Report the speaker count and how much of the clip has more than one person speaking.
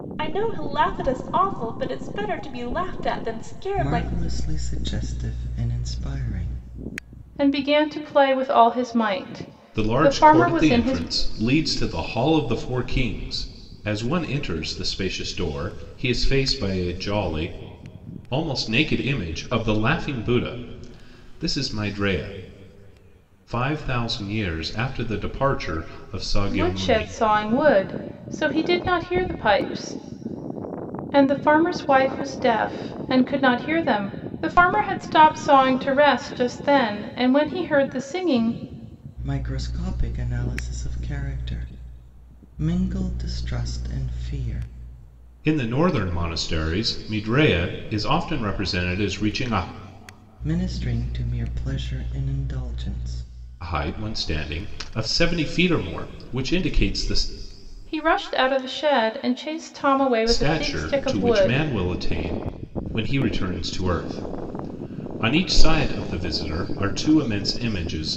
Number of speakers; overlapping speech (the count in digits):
4, about 6%